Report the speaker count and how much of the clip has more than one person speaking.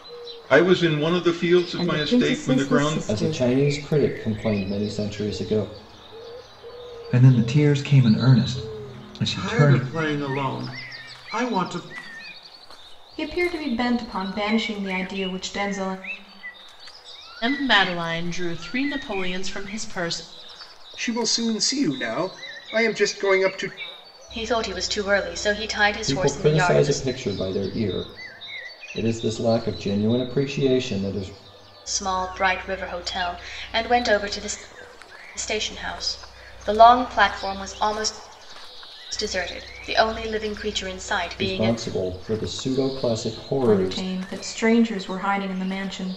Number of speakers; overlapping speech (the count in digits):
9, about 9%